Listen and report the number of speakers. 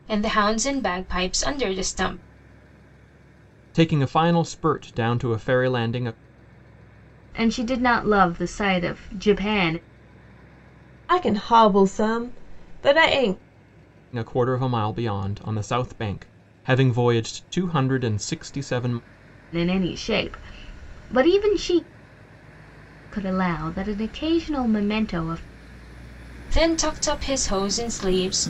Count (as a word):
four